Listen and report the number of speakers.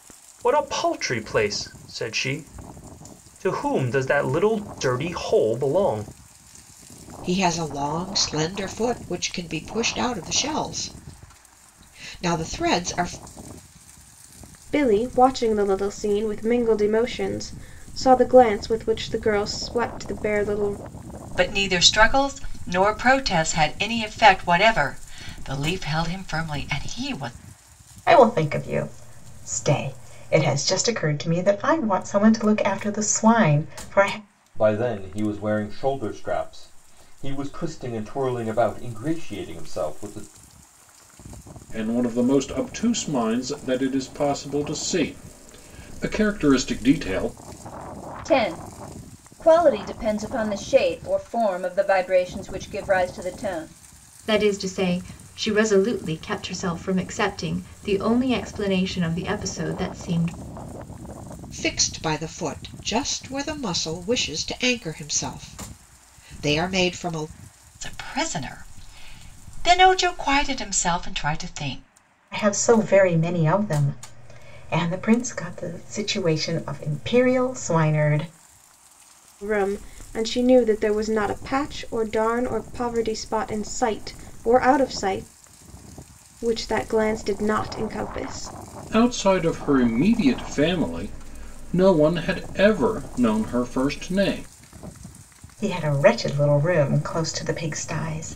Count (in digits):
9